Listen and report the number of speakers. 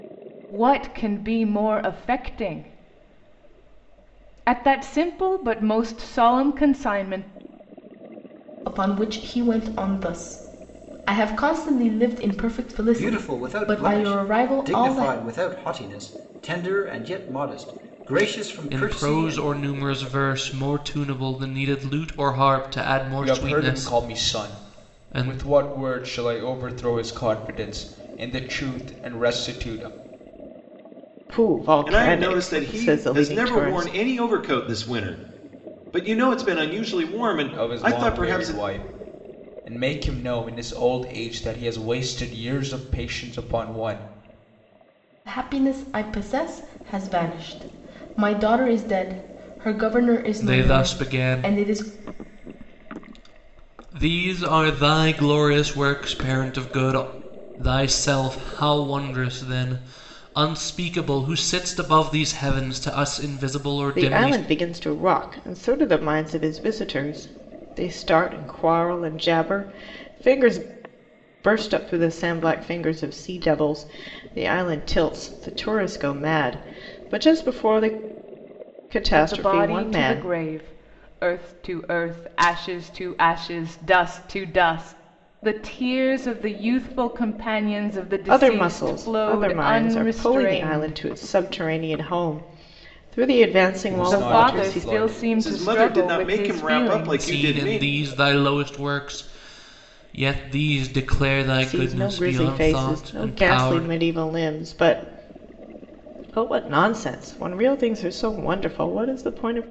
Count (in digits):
7